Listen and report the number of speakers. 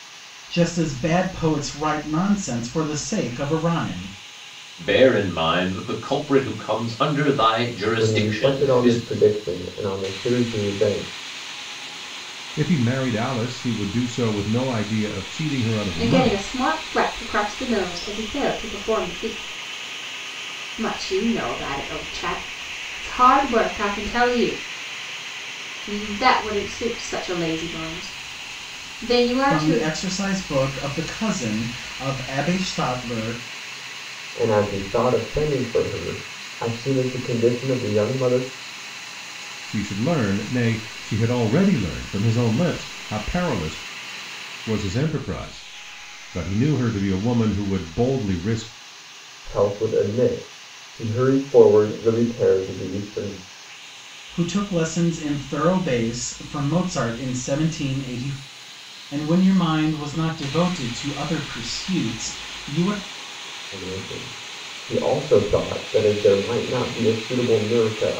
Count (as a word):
five